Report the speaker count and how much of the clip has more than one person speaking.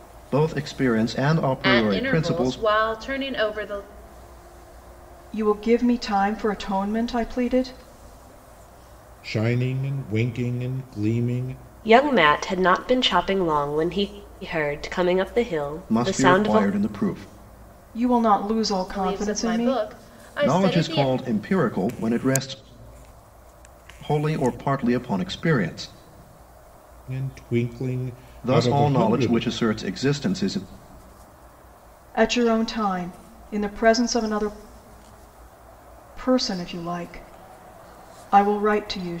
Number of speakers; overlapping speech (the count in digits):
5, about 11%